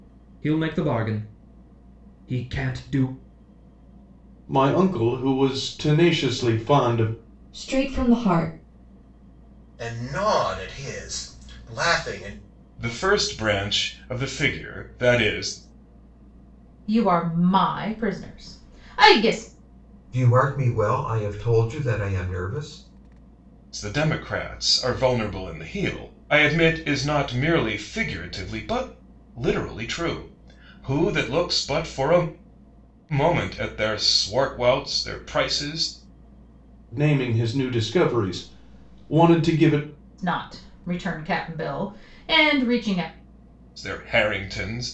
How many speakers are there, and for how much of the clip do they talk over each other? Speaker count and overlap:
seven, no overlap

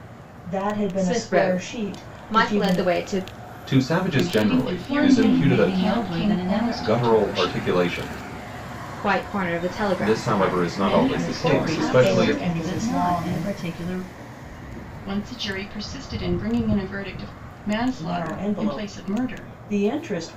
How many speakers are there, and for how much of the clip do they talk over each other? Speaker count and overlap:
five, about 53%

